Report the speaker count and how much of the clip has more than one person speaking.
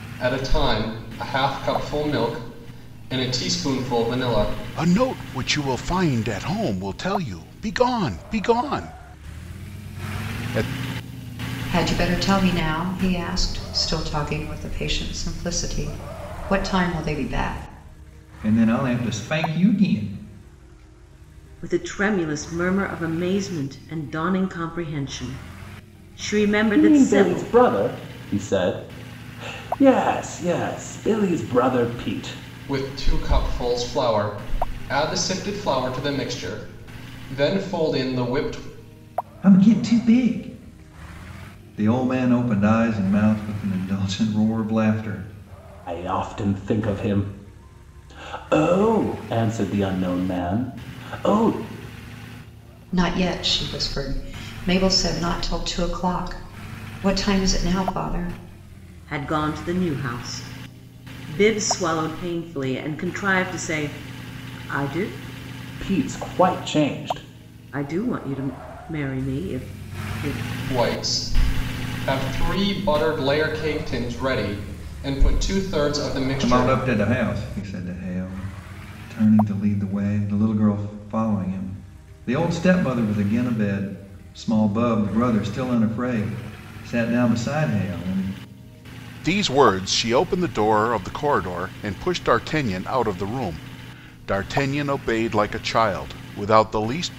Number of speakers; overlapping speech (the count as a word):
six, about 1%